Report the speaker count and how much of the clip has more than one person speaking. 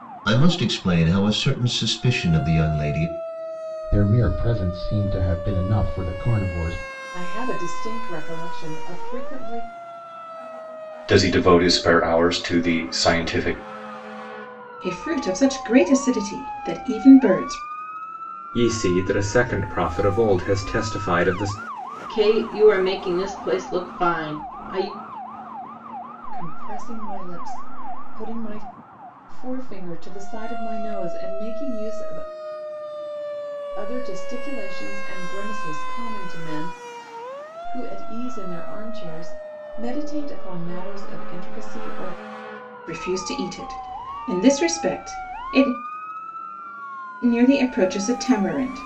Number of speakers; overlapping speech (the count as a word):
seven, no overlap